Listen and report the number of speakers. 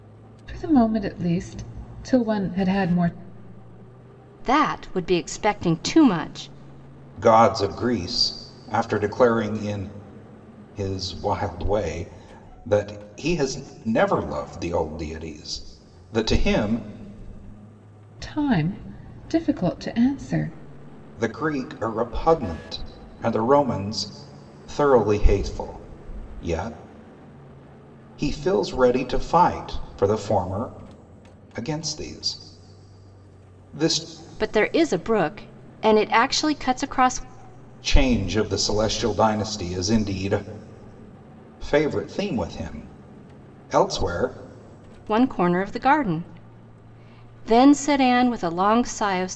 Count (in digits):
3